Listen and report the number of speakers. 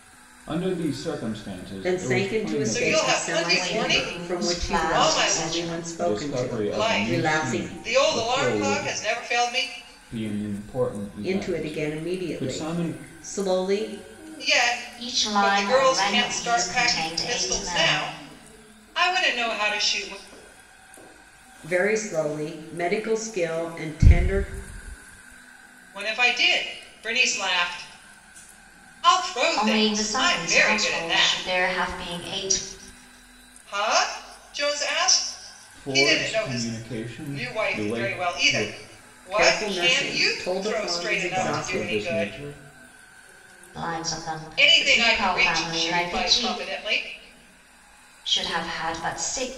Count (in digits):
4